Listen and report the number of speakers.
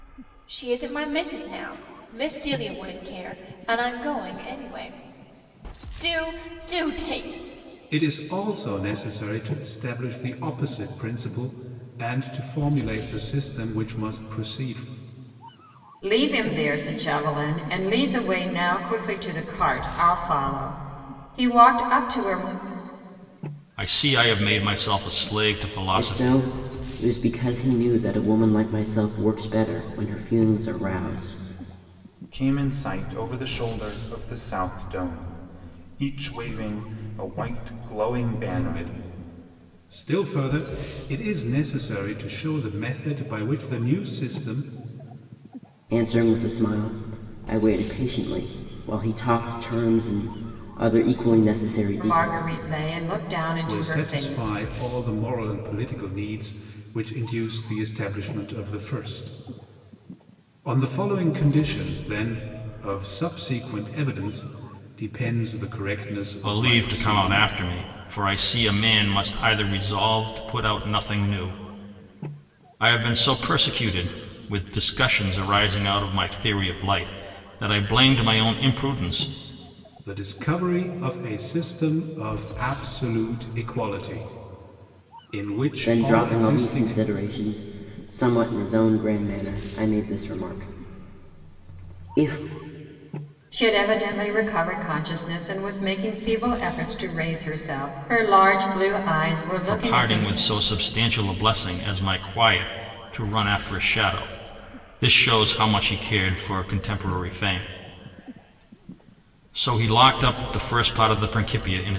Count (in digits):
6